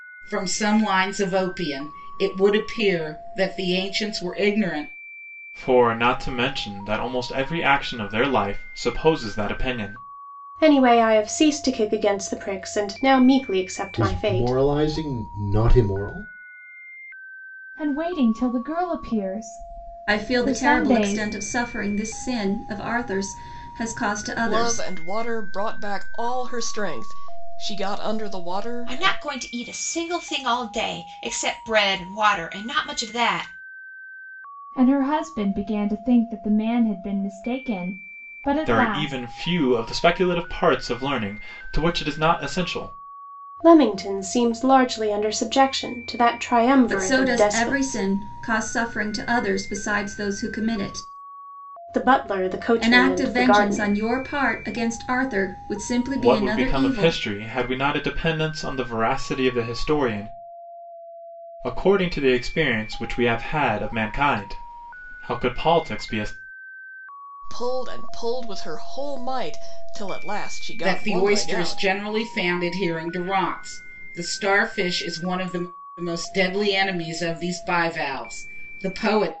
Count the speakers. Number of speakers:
8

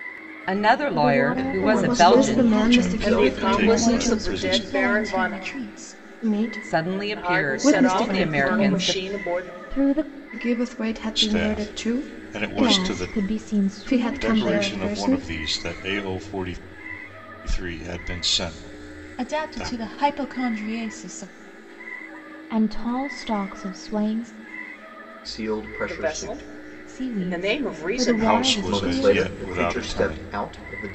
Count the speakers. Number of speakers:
7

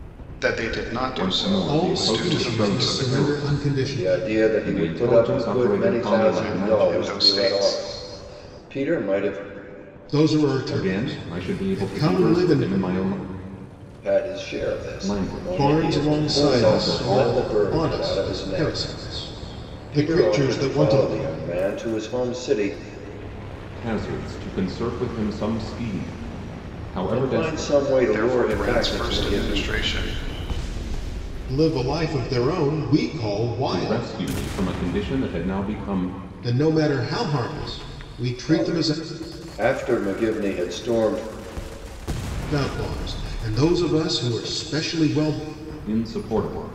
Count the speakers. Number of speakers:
4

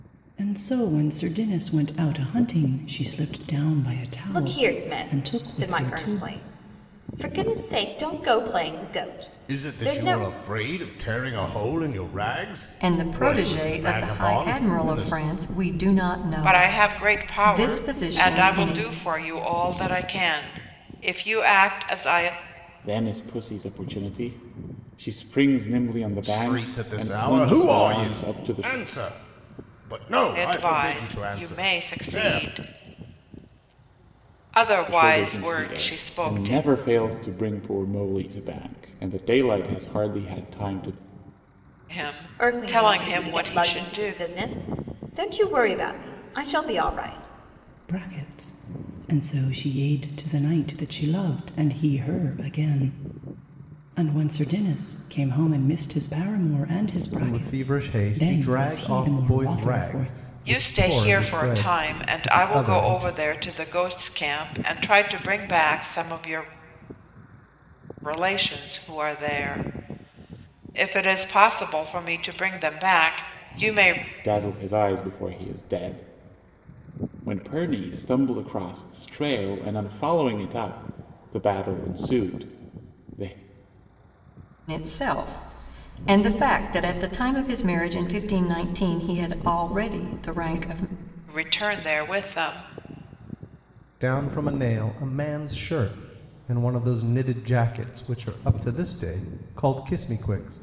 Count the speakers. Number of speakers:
6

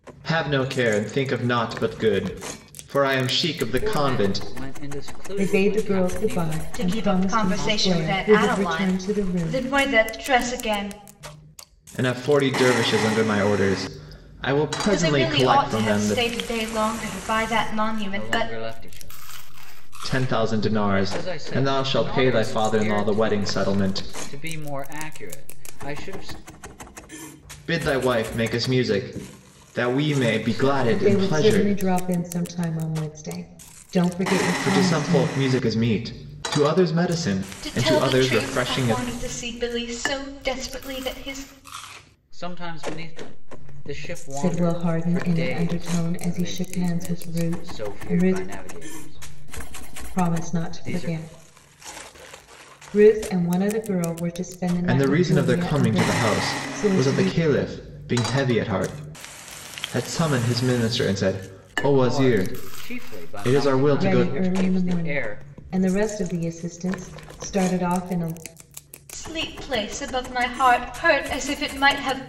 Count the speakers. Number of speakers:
4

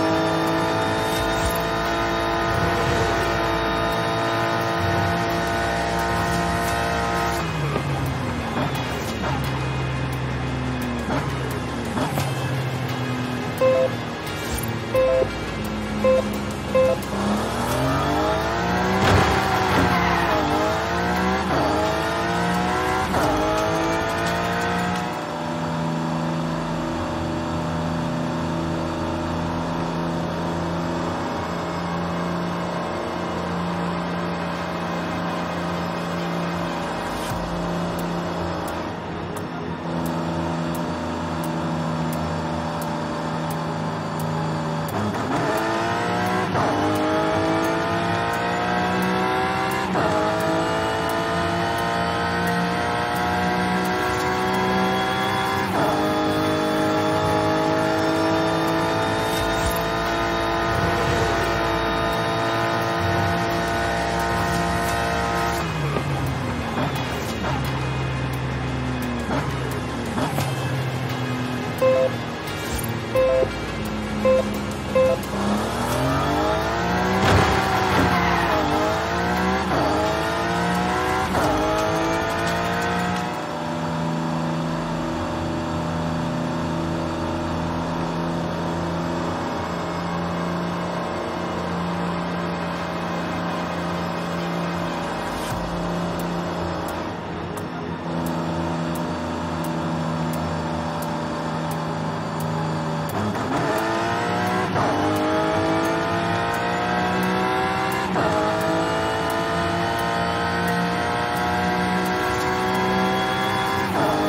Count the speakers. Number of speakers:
0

